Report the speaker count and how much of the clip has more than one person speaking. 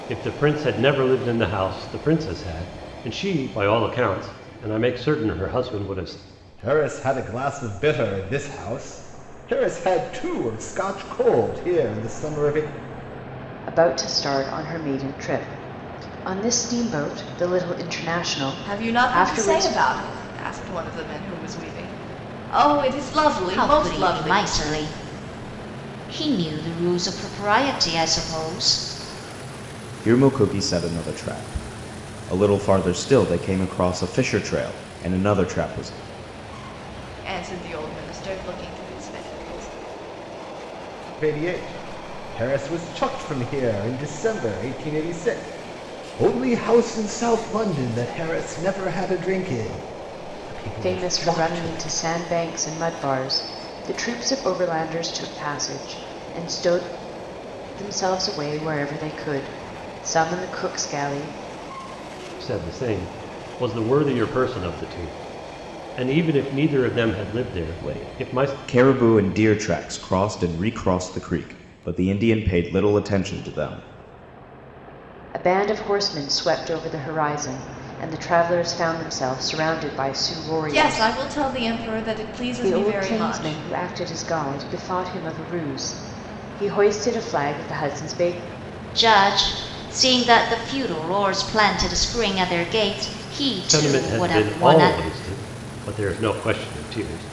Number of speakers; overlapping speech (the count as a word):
six, about 7%